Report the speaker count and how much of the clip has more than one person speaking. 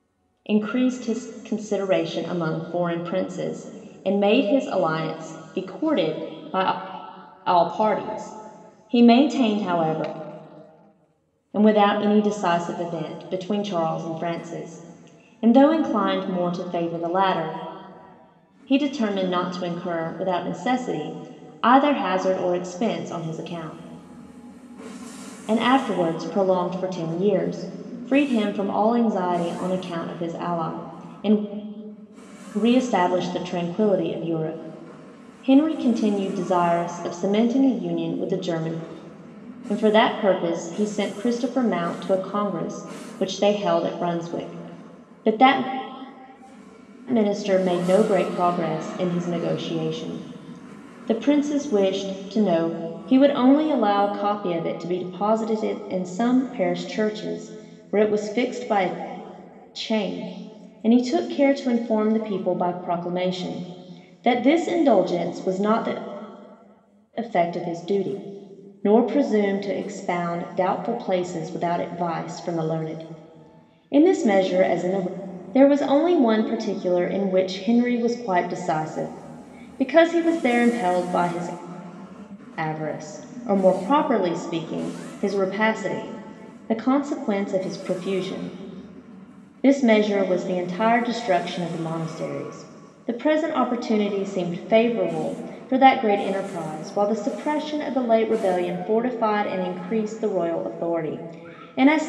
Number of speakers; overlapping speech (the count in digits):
1, no overlap